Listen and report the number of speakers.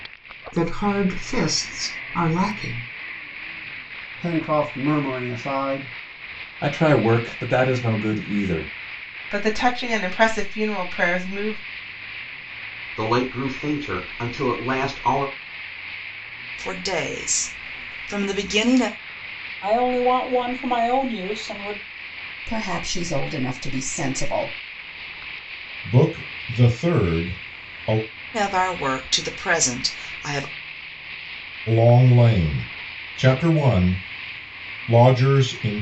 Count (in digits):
9